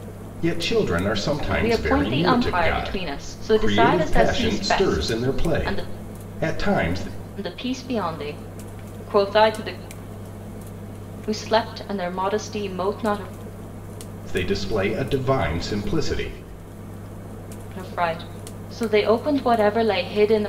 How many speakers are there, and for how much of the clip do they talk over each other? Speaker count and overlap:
two, about 22%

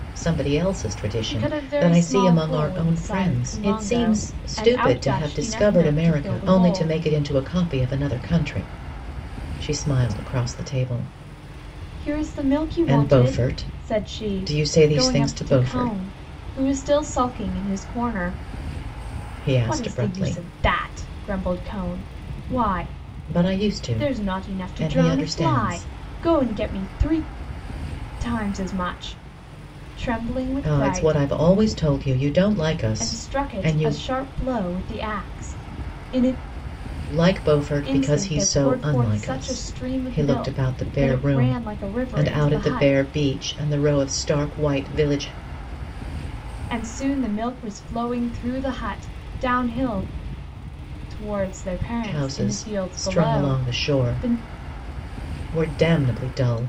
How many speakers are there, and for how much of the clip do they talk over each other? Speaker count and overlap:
two, about 35%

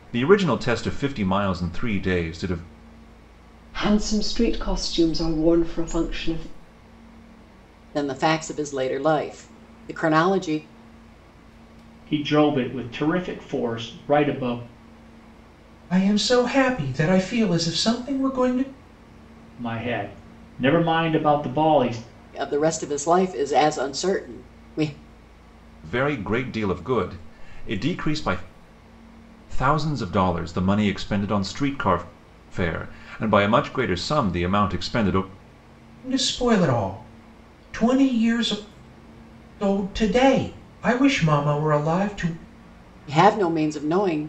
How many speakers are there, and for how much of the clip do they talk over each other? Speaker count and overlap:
five, no overlap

